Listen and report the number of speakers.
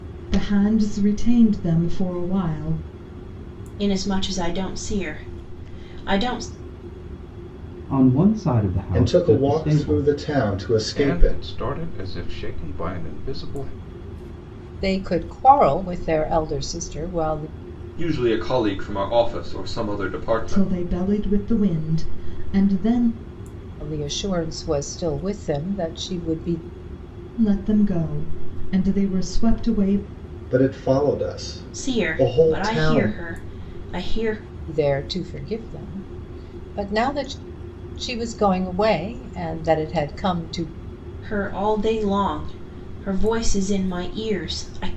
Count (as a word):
seven